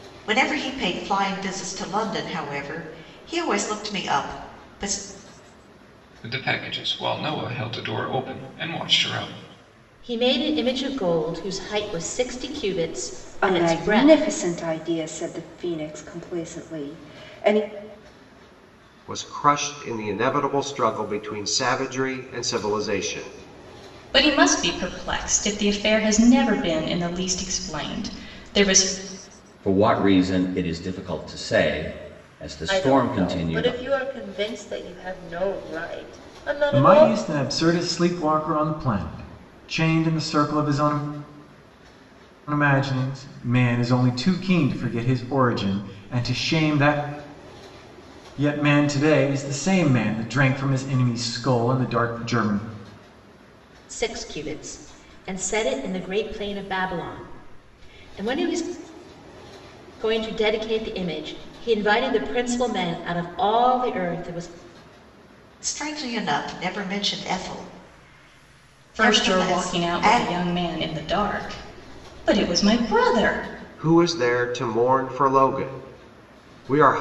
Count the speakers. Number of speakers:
9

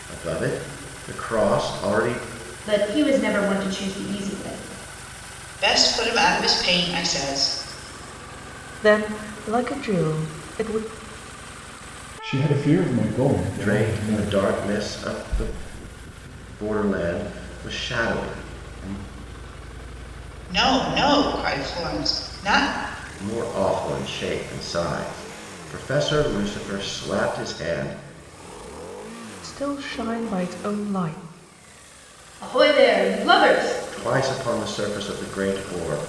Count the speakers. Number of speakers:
5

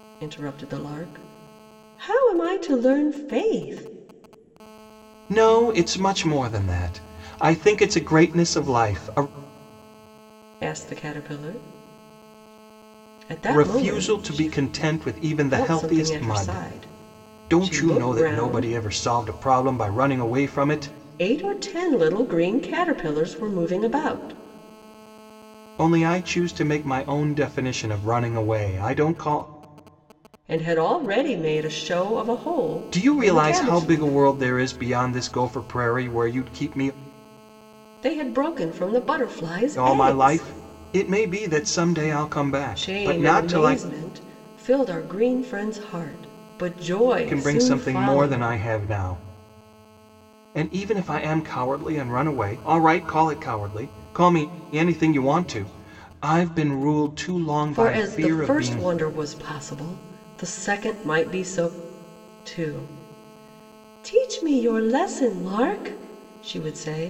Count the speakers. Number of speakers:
2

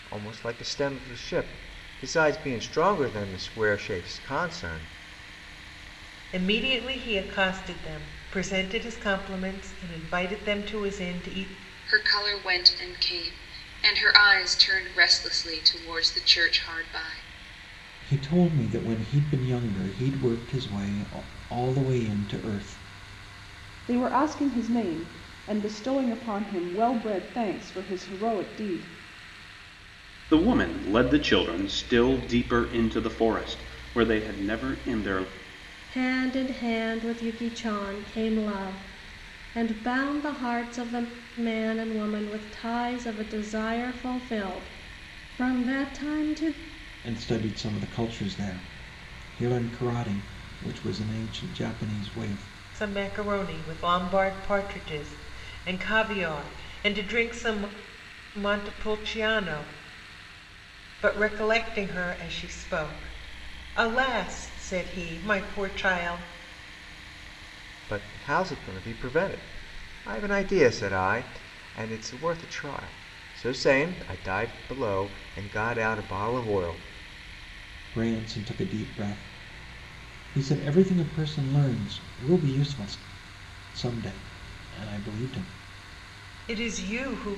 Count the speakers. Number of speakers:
7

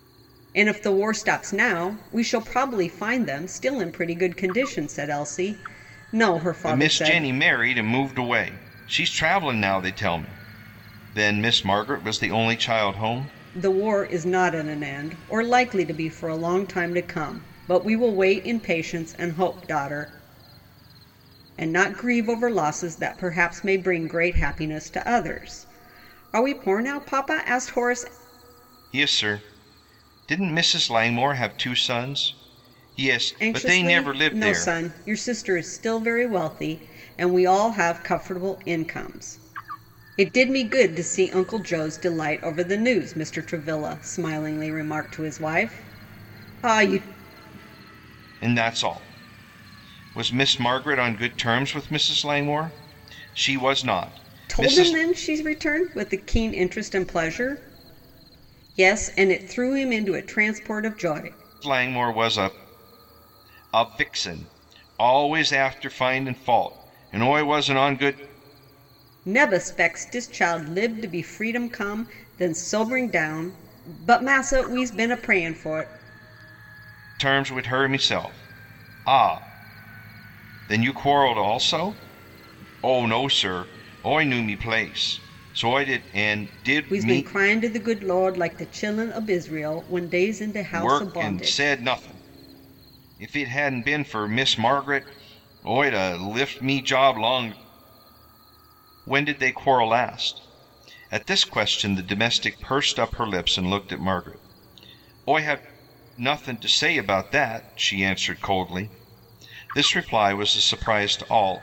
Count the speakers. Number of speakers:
2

